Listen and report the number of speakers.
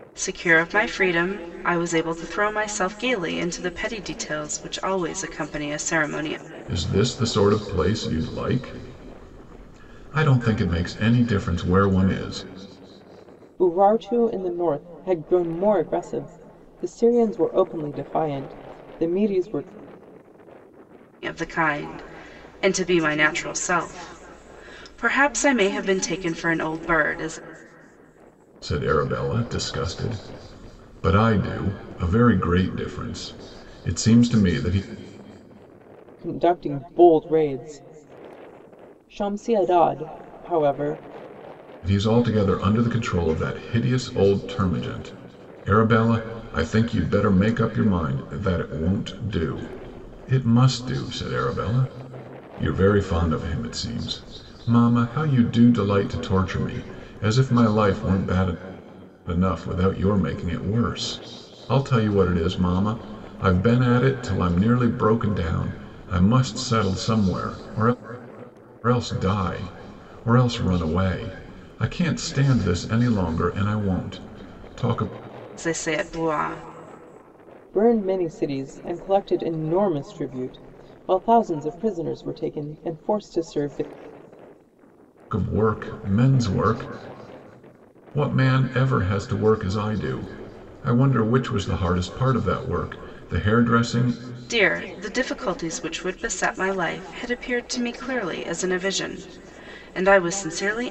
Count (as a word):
three